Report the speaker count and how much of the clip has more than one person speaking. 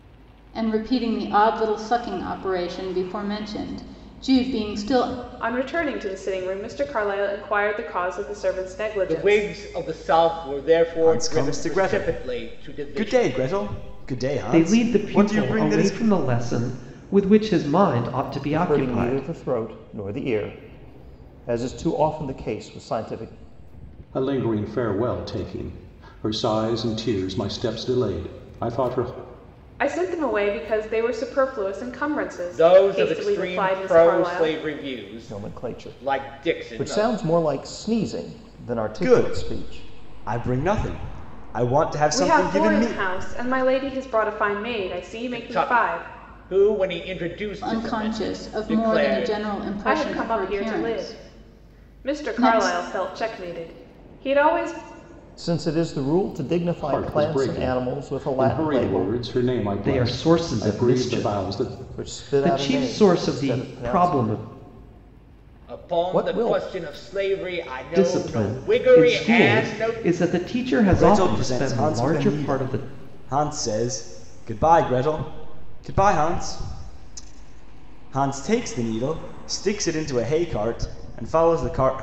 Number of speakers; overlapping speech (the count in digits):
7, about 35%